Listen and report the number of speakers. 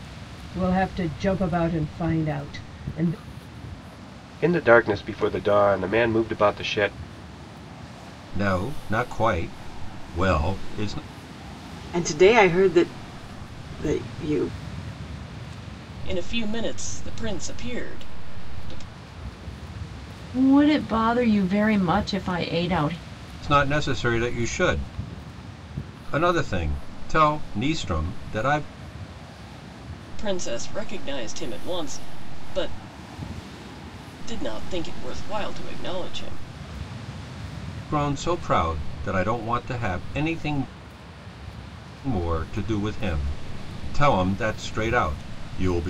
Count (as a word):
six